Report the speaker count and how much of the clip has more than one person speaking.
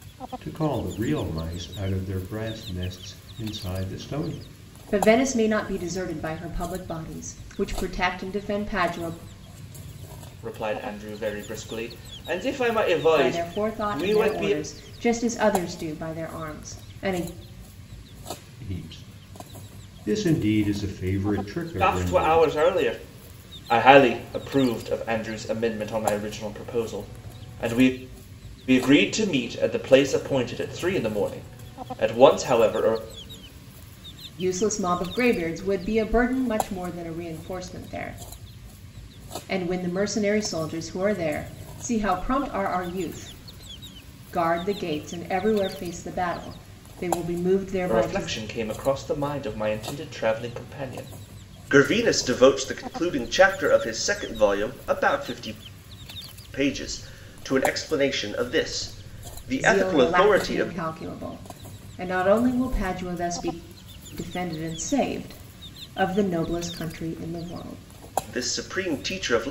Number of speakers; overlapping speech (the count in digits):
3, about 5%